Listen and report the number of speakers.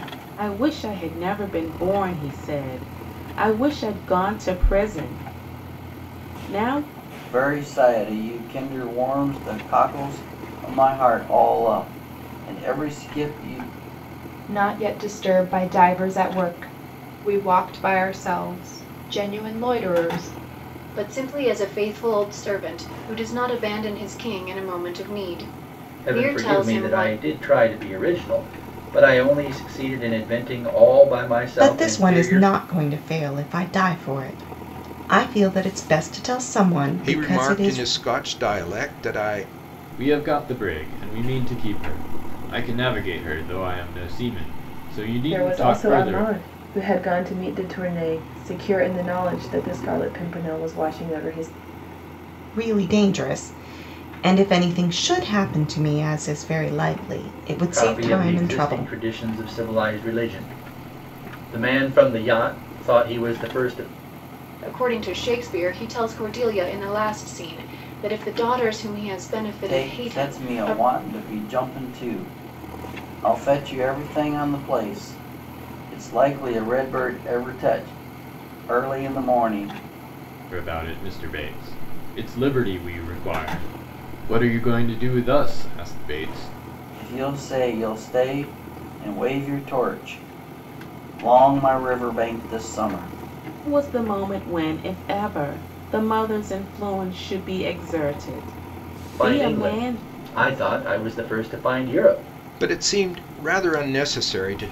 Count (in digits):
9